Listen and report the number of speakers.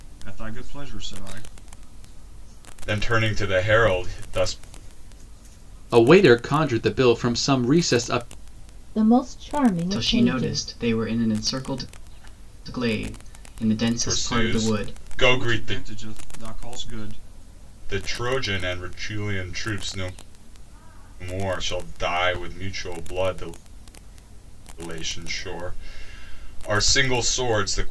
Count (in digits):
5